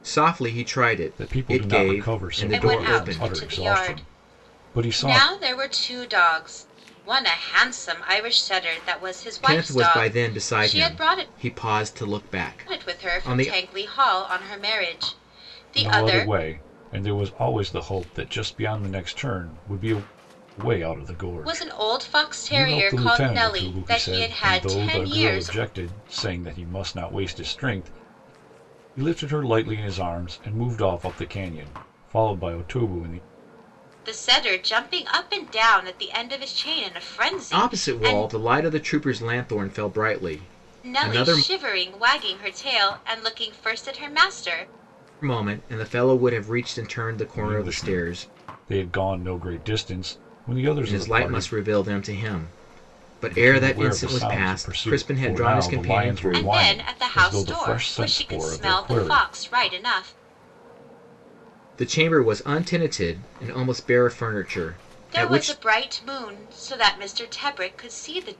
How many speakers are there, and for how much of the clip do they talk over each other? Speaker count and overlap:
3, about 31%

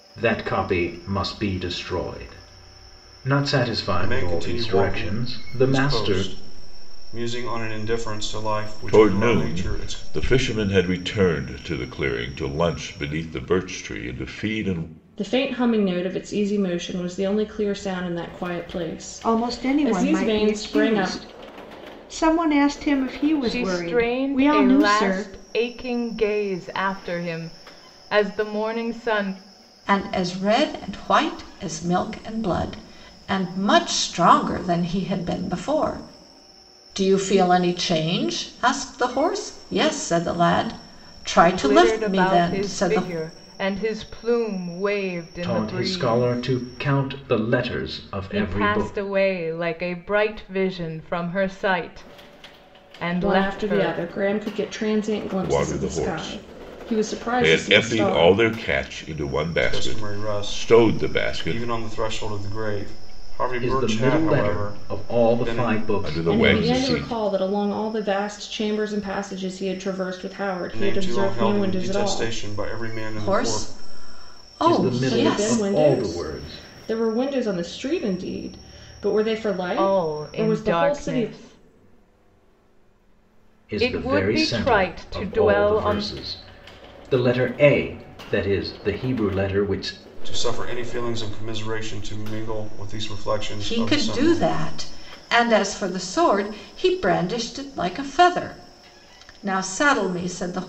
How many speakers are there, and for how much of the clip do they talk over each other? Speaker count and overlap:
7, about 29%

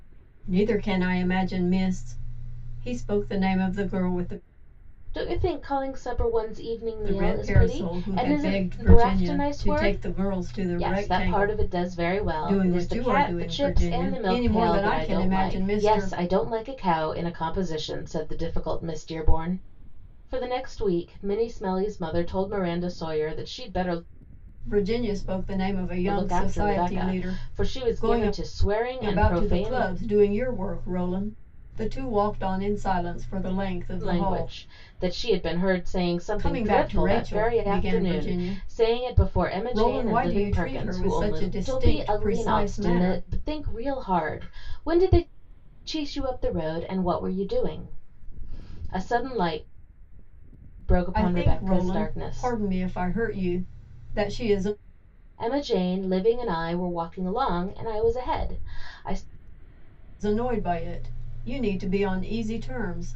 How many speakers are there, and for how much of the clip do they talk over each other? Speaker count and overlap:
2, about 31%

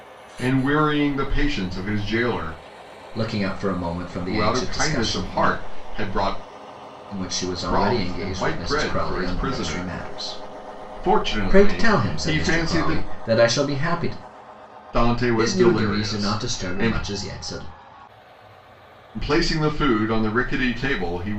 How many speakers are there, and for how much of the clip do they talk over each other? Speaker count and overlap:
2, about 35%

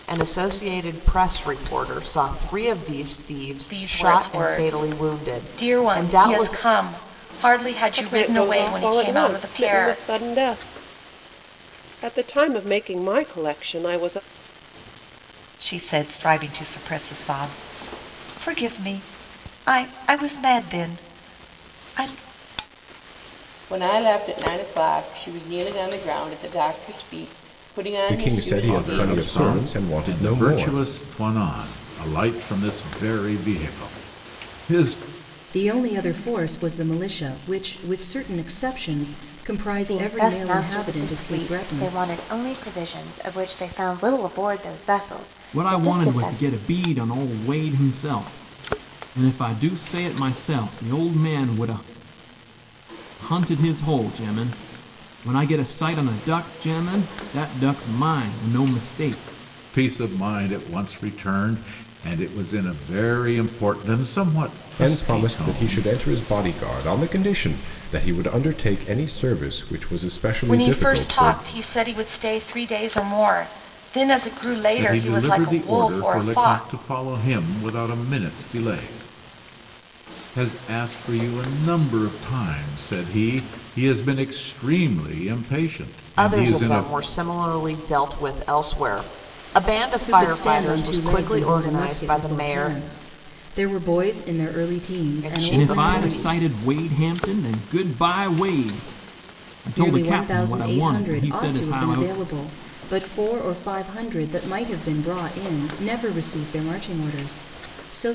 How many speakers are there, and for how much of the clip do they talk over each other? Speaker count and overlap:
10, about 21%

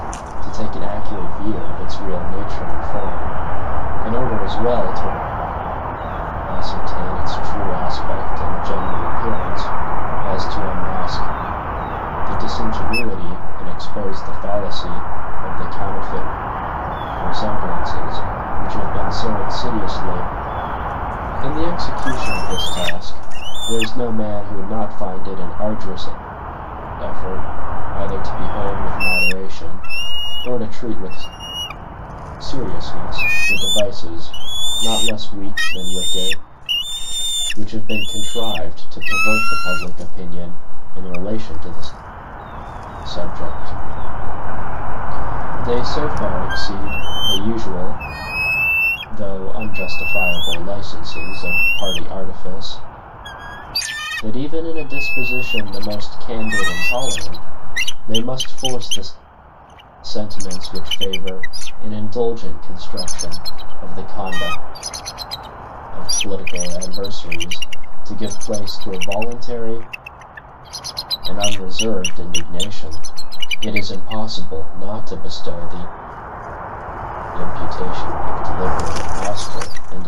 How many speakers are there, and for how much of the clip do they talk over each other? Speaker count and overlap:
1, no overlap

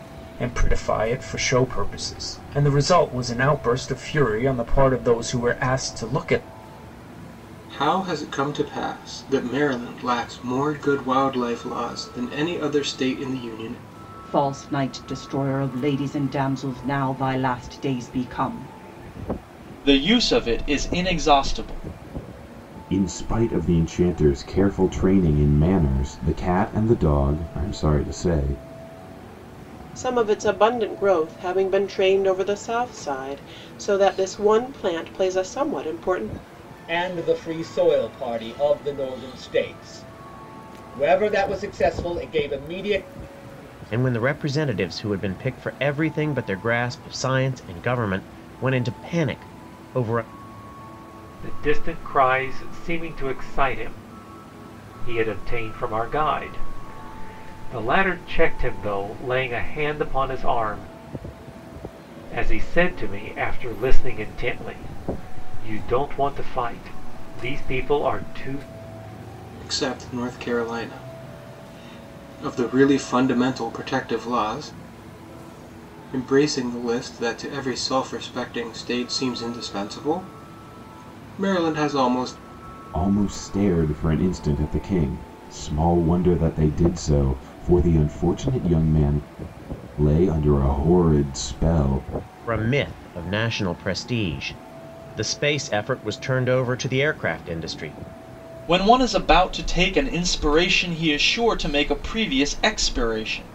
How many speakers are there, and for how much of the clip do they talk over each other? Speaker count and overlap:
9, no overlap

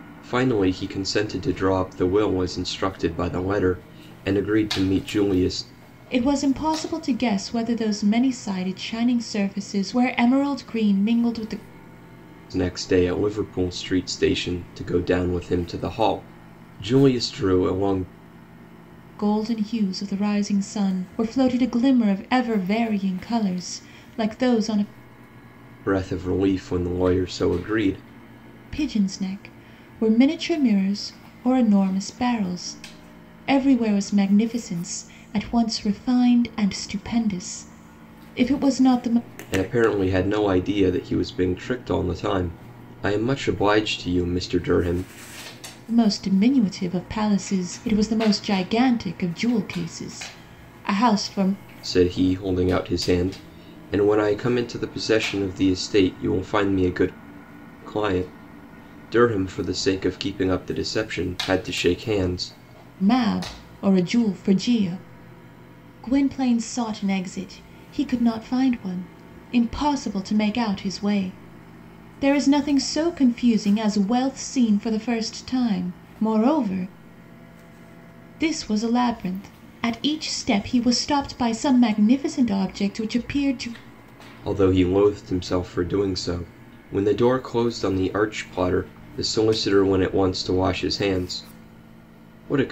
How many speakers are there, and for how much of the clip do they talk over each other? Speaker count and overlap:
2, no overlap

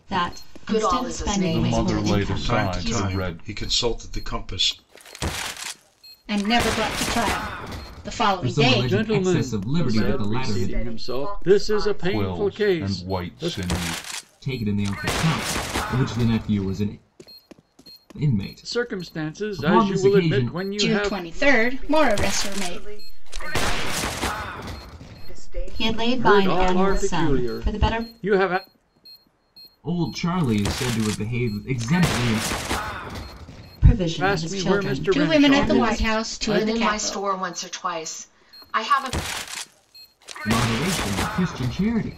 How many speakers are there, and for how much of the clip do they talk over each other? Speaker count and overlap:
8, about 42%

